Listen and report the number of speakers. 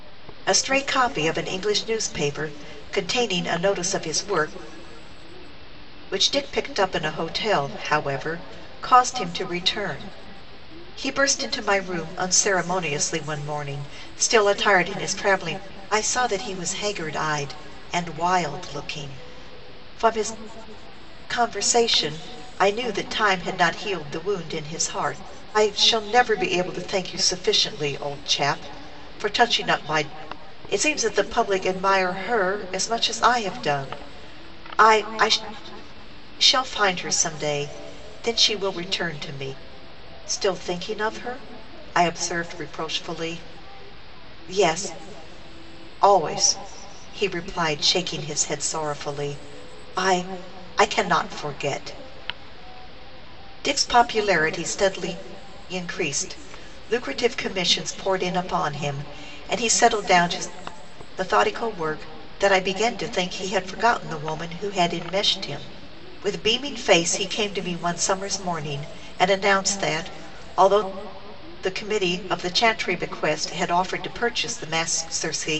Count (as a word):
one